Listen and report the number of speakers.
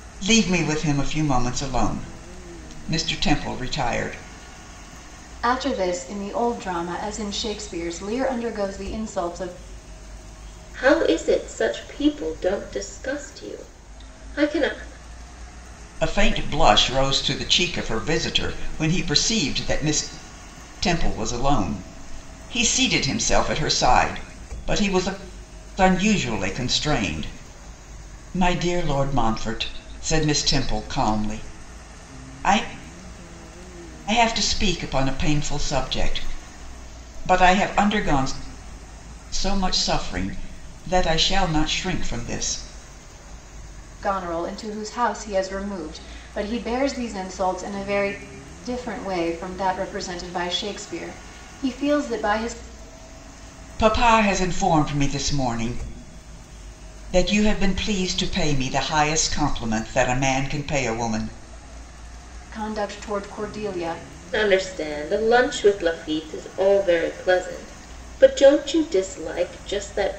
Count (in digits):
3